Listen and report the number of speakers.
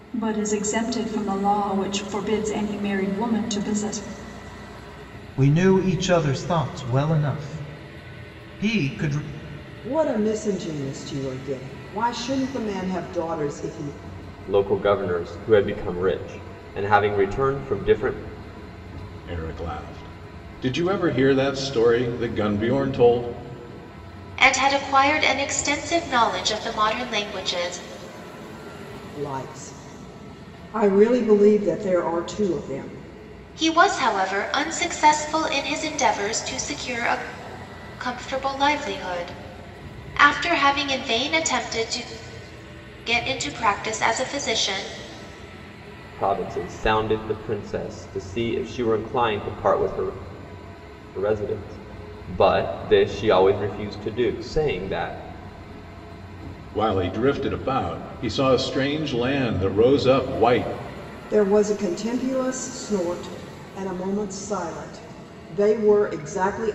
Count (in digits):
6